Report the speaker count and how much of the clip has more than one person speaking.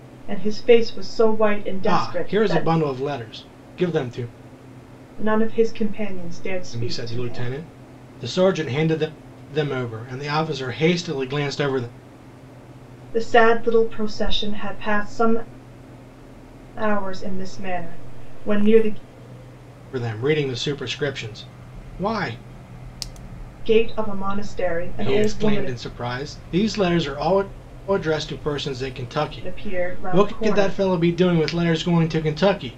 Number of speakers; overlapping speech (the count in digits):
2, about 11%